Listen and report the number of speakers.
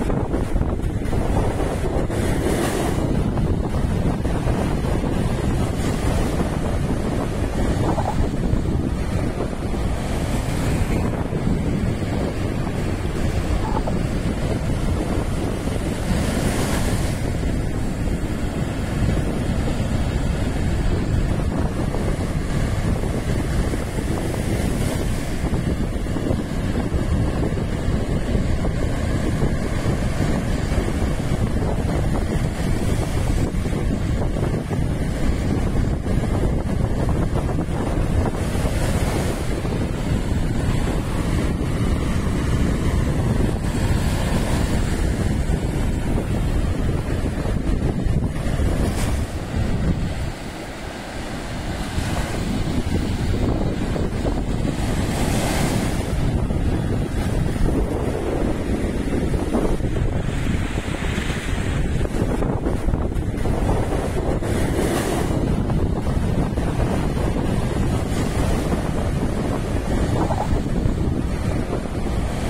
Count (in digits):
0